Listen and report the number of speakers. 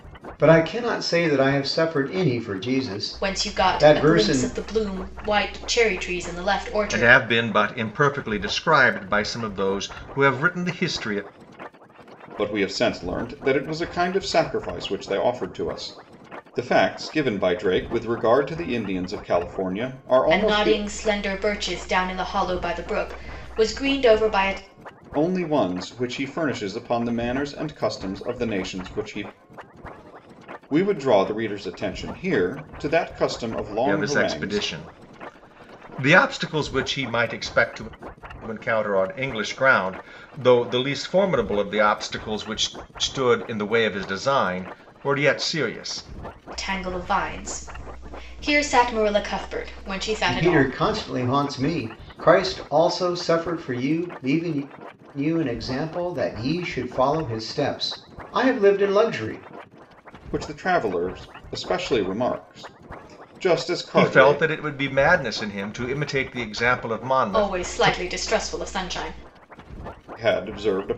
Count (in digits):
4